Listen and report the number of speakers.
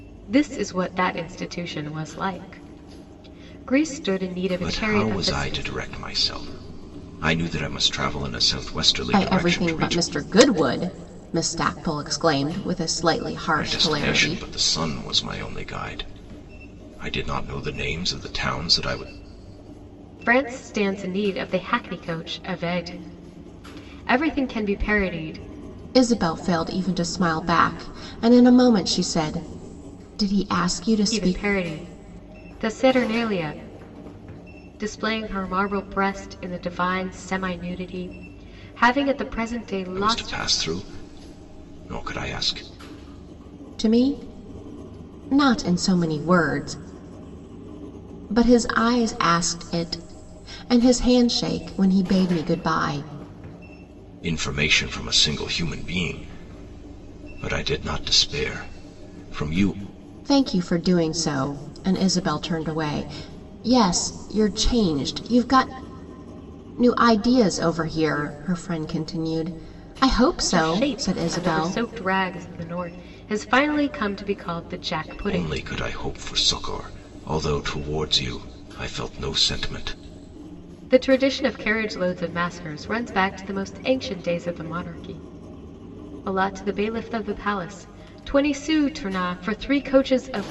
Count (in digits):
3